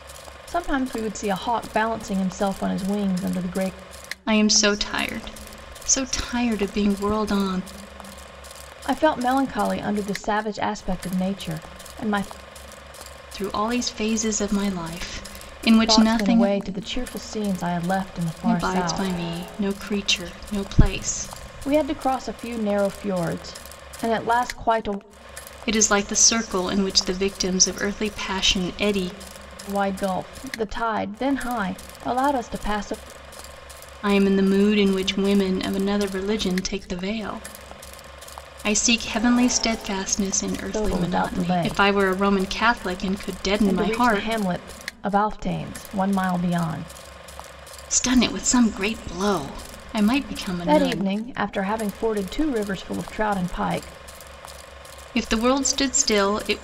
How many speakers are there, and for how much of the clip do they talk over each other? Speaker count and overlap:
two, about 7%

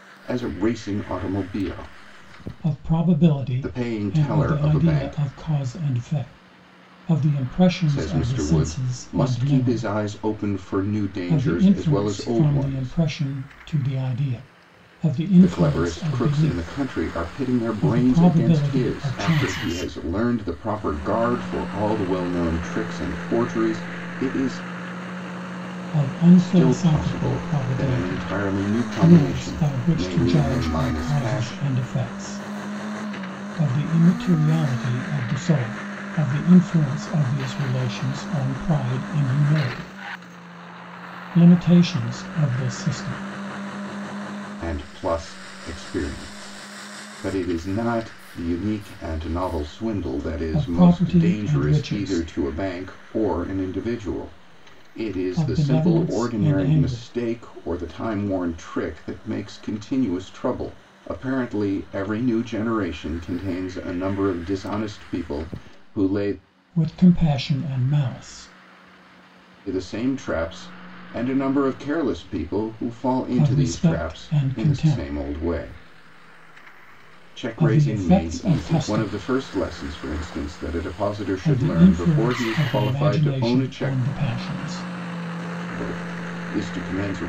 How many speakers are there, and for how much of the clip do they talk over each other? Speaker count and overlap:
two, about 28%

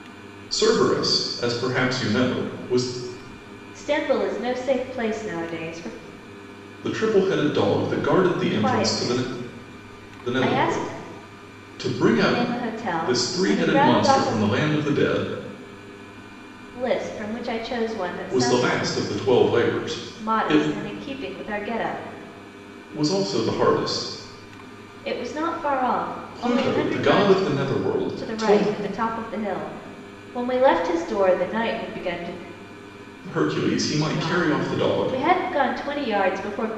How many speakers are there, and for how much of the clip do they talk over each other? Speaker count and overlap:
two, about 20%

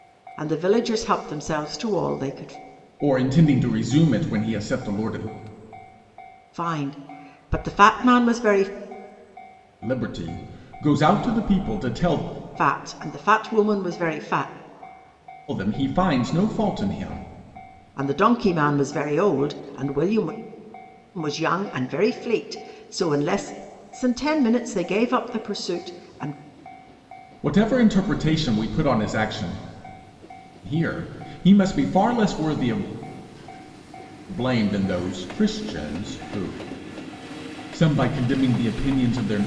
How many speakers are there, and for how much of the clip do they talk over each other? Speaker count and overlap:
two, no overlap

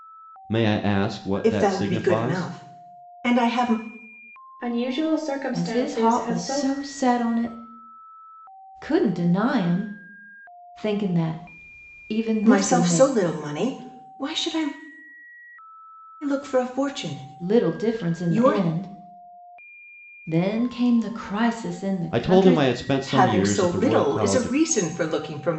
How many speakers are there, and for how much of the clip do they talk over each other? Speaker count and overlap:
four, about 25%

